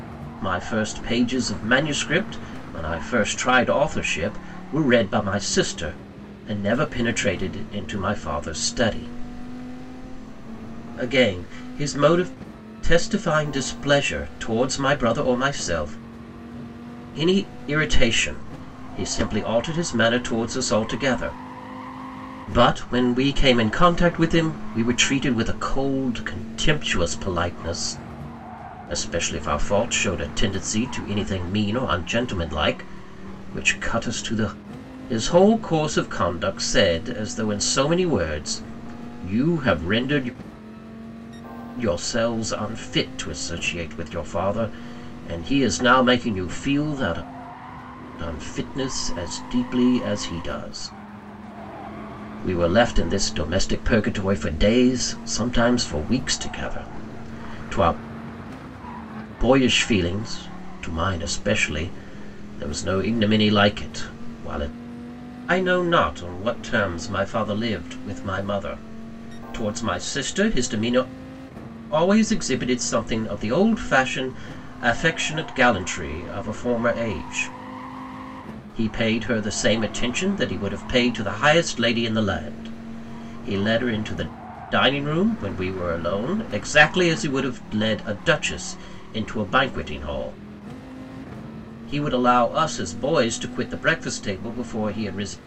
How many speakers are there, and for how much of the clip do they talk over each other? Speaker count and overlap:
one, no overlap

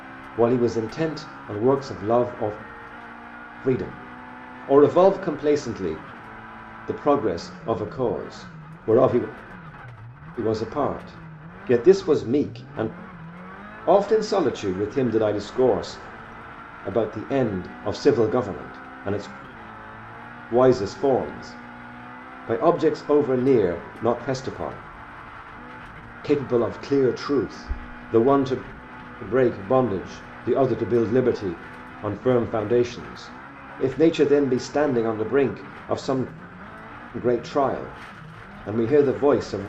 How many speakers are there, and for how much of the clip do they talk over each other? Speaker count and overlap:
one, no overlap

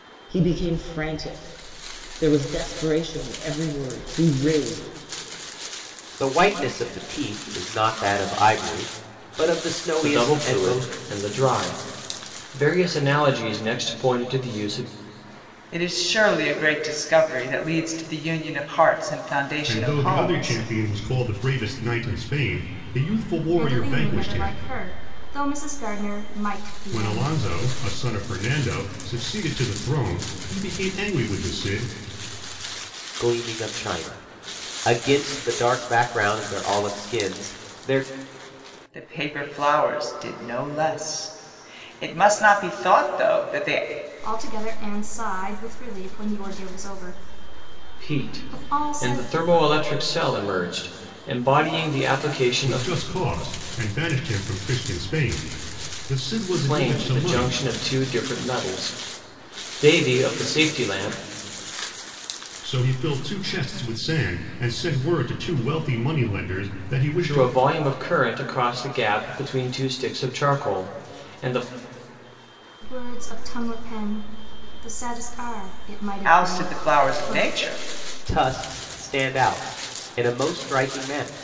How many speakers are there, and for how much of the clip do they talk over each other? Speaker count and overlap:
six, about 10%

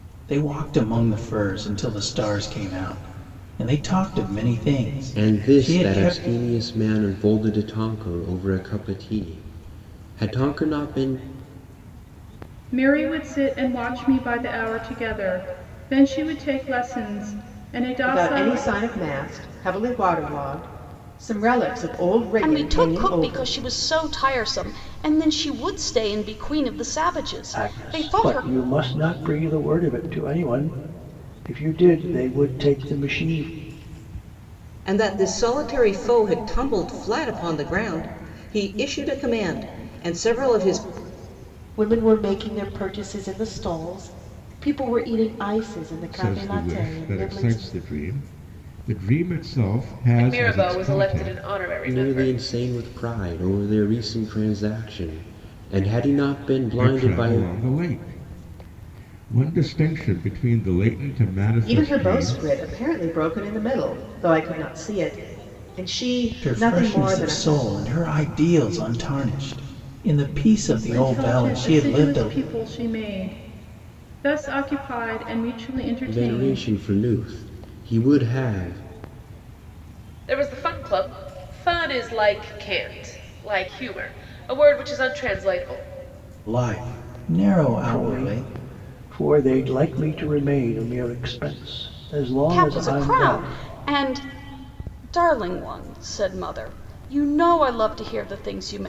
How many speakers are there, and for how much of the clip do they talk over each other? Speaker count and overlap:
ten, about 14%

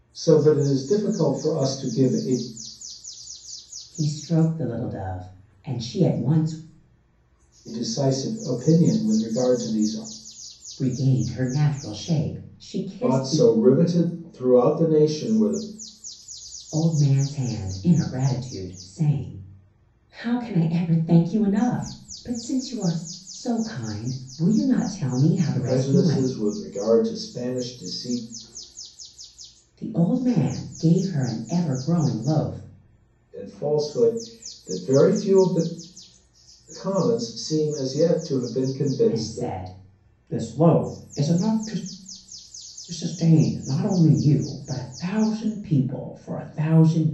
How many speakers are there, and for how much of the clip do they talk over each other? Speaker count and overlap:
two, about 4%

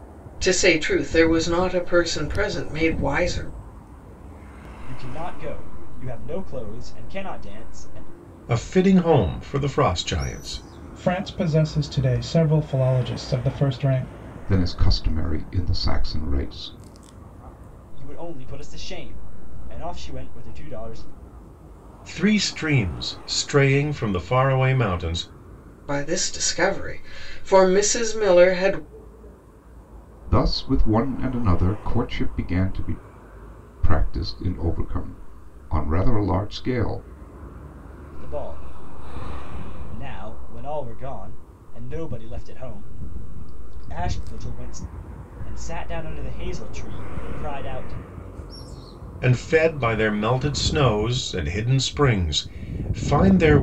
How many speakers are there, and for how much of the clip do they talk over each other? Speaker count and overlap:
five, no overlap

